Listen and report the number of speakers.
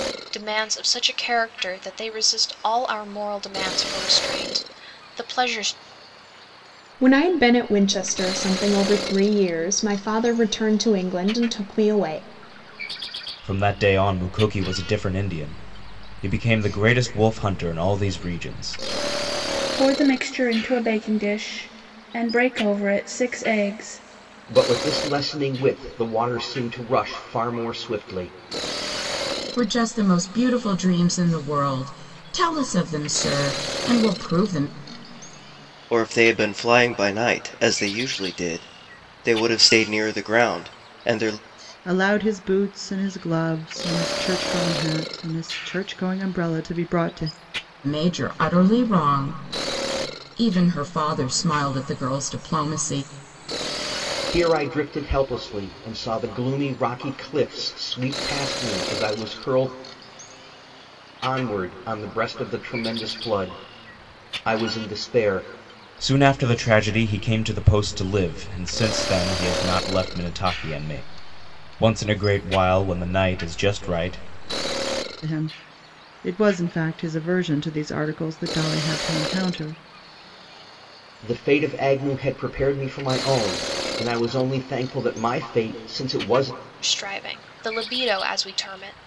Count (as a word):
eight